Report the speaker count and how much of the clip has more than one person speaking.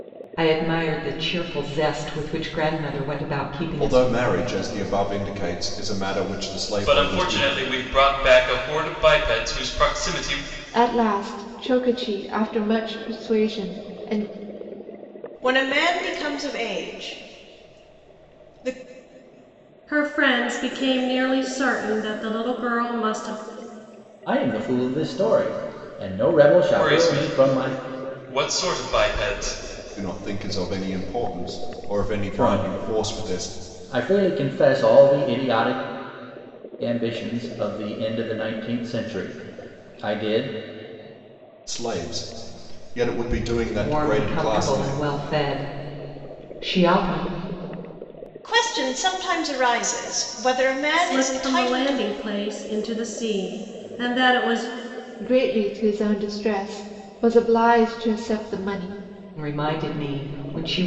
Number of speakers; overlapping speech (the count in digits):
7, about 9%